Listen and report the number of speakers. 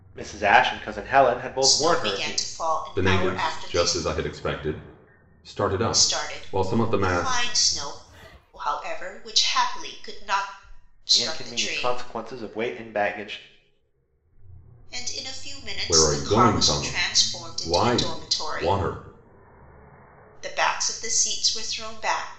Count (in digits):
3